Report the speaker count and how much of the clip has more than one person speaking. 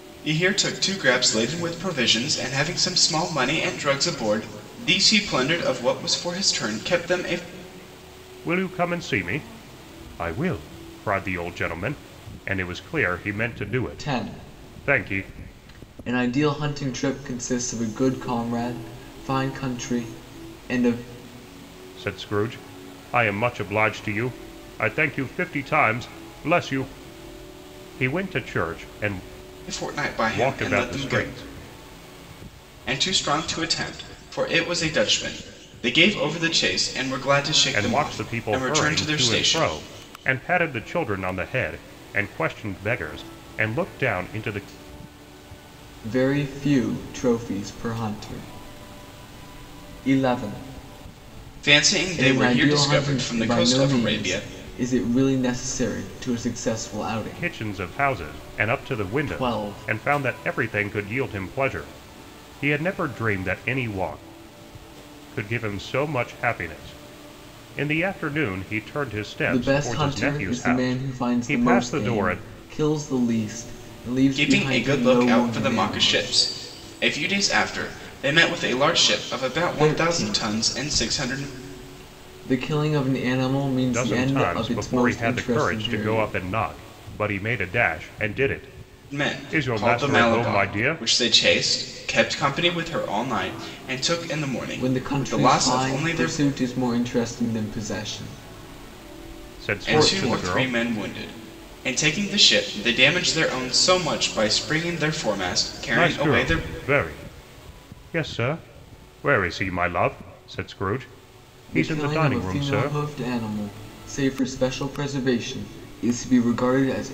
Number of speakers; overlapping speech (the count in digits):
3, about 22%